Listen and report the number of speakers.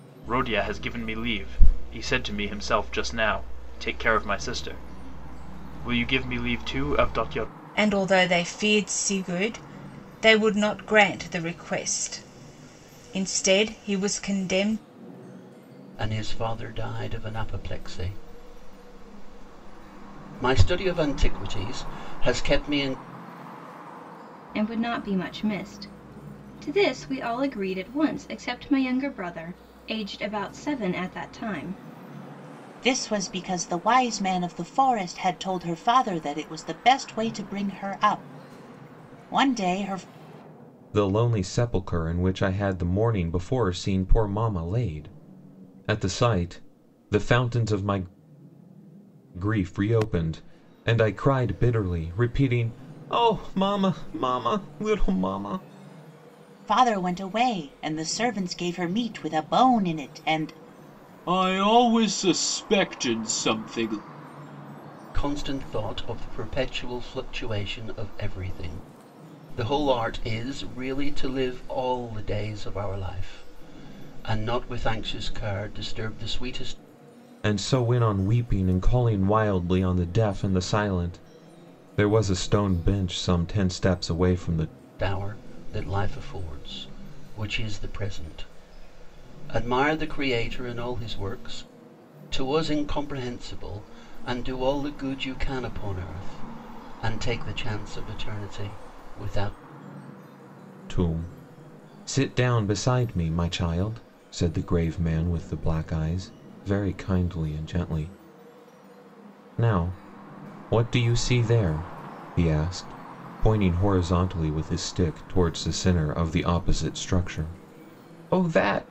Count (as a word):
six